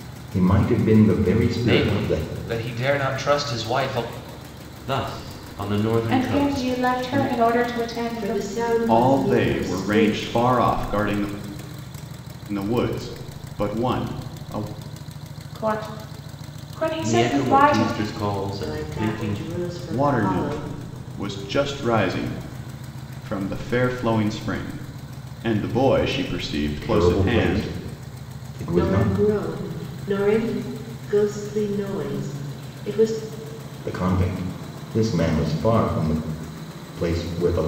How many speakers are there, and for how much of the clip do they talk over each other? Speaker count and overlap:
6, about 20%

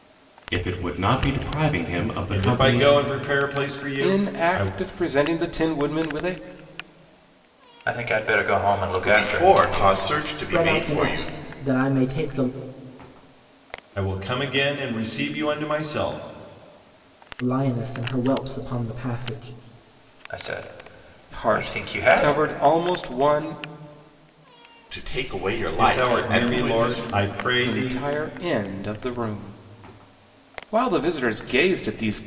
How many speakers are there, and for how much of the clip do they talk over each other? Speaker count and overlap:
6, about 19%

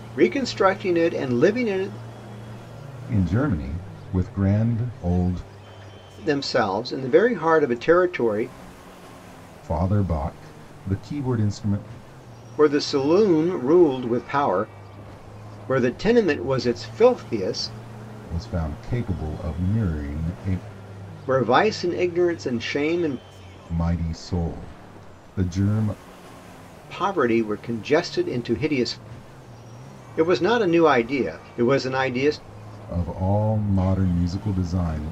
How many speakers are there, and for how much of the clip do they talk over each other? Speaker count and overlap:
2, no overlap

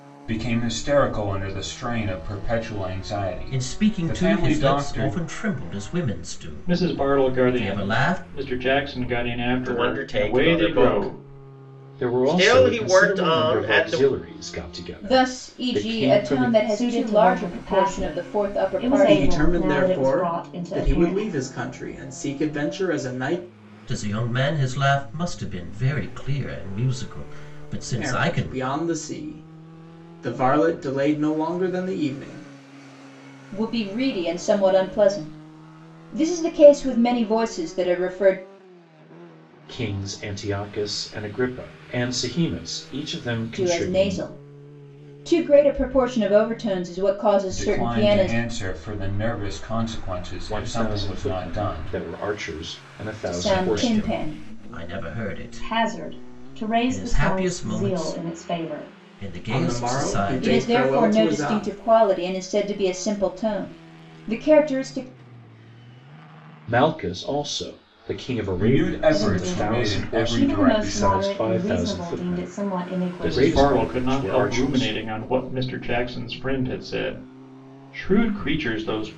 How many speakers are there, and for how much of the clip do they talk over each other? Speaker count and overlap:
8, about 38%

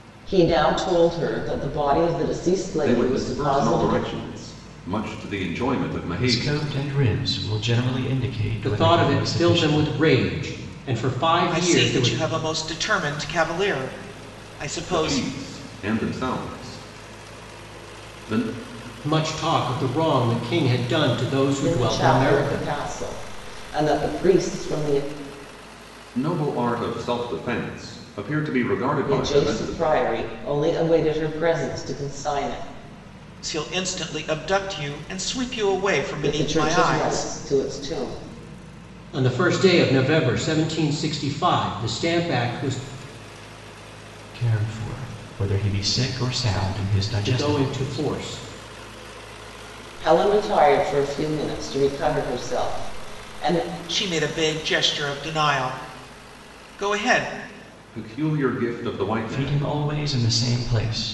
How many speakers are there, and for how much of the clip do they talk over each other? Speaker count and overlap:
5, about 14%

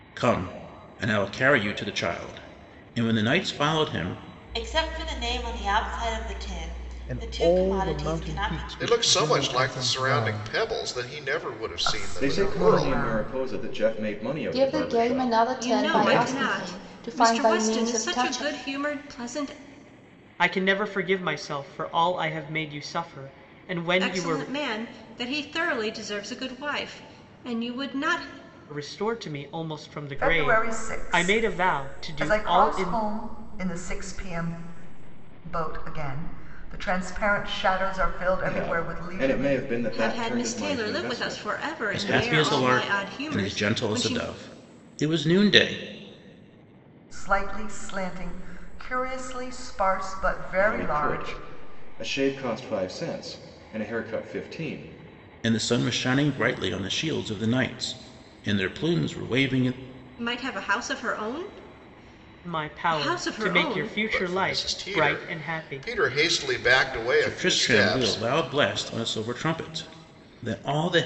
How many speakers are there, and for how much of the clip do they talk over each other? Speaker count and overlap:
9, about 33%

